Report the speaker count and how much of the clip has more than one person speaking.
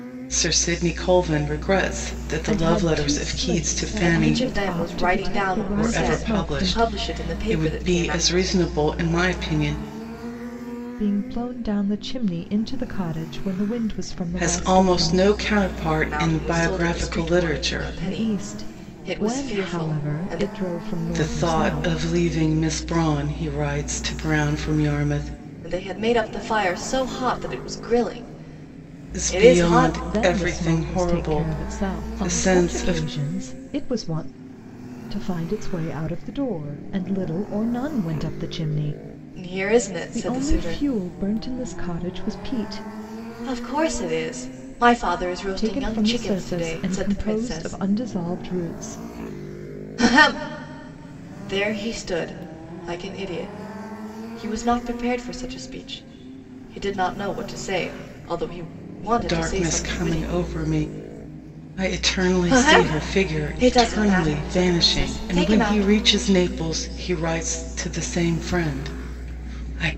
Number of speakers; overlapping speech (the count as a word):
three, about 34%